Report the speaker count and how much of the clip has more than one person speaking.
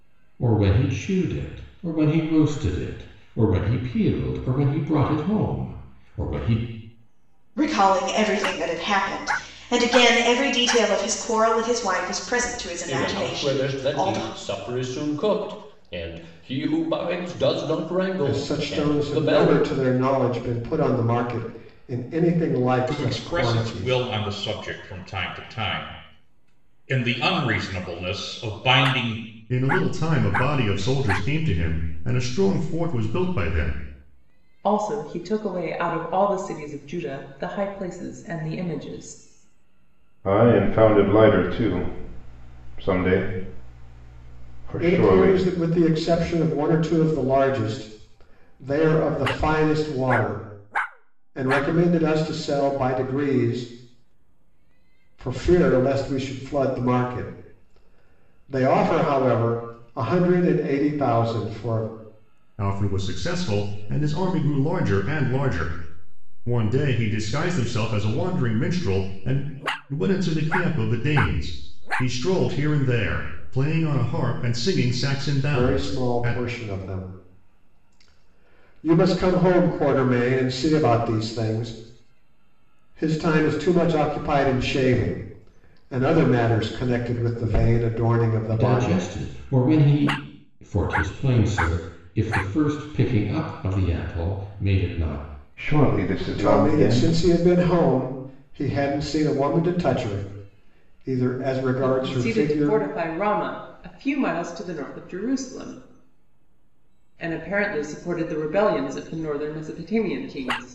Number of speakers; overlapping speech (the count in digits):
8, about 7%